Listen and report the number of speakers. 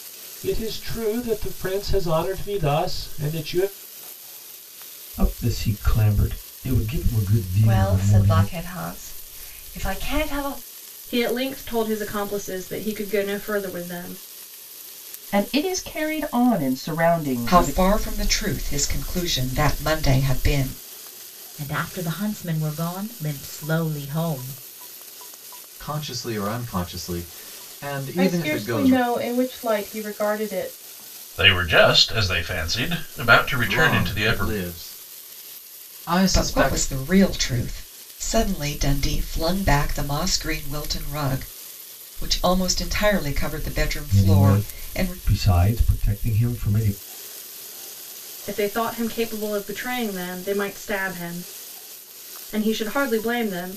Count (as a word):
ten